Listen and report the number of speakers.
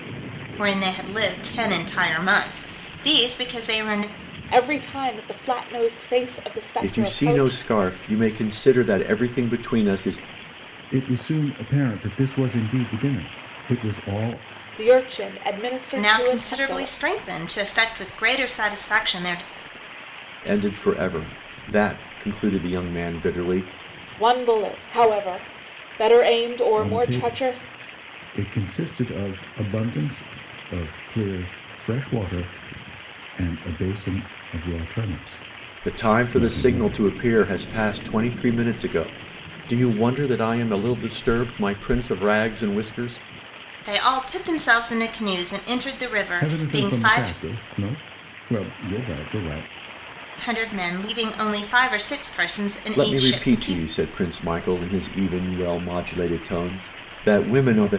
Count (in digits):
4